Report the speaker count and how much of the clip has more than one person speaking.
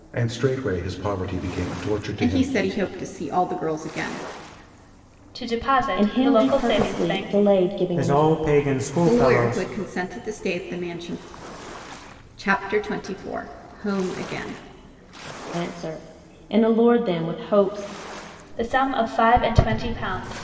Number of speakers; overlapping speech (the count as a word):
five, about 14%